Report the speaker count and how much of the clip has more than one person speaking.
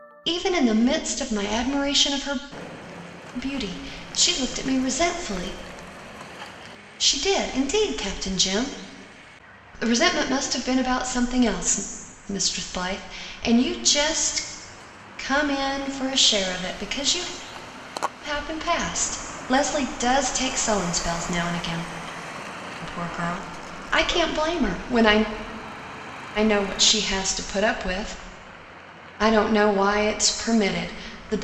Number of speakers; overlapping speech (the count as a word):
one, no overlap